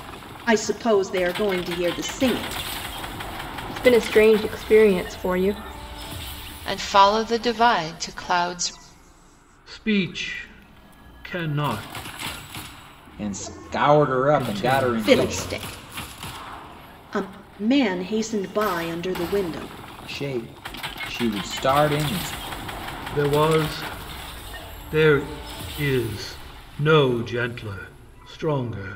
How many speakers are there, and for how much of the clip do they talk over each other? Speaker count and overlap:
5, about 5%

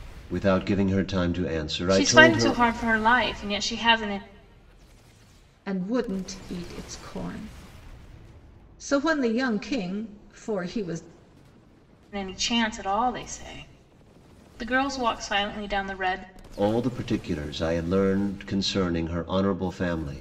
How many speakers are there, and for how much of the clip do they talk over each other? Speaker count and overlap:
3, about 4%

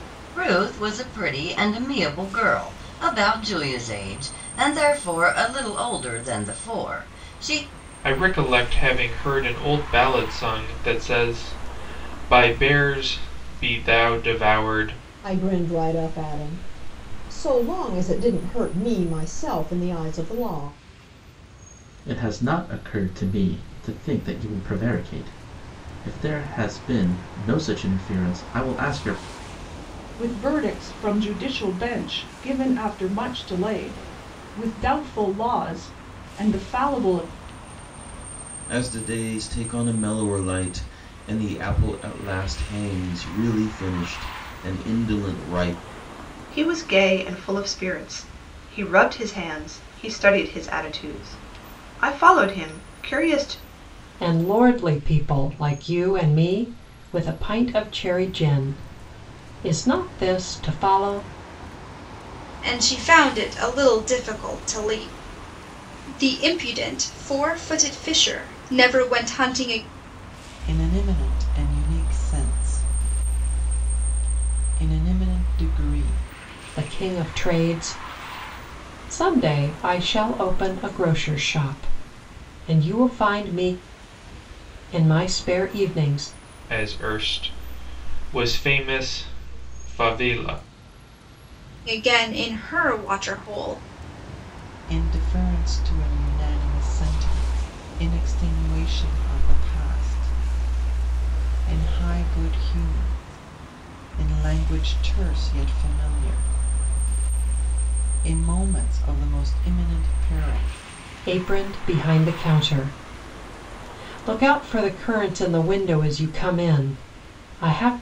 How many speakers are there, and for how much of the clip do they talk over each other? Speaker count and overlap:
10, no overlap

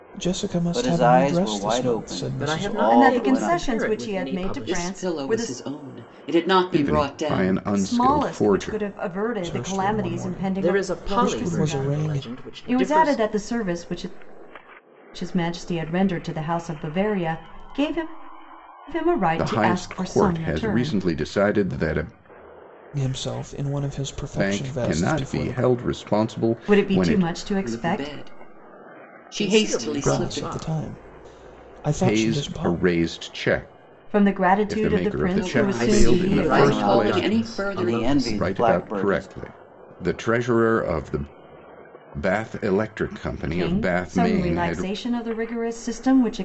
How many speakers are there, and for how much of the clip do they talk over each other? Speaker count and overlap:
6, about 50%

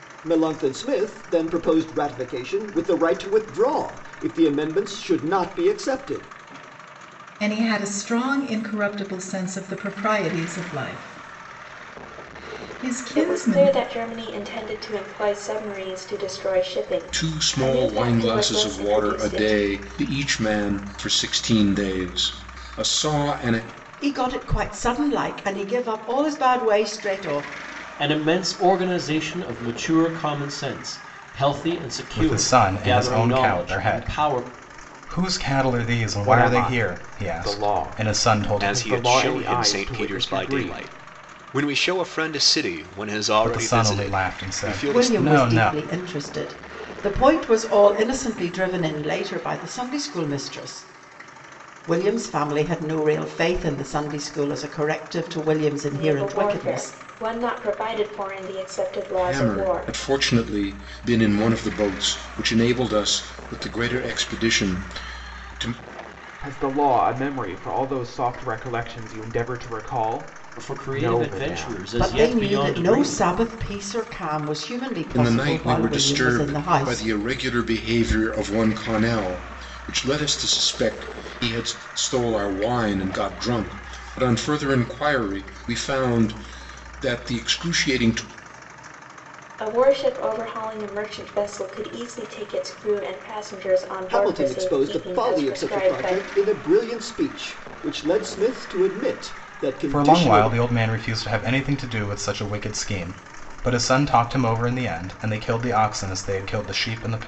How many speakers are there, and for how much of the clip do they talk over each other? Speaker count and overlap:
9, about 21%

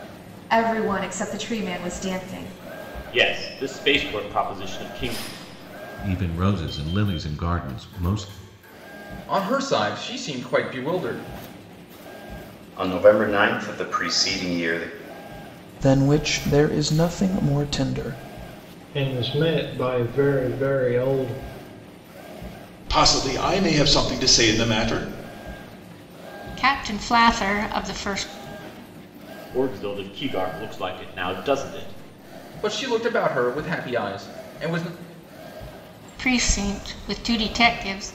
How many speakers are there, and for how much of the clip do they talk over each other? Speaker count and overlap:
9, no overlap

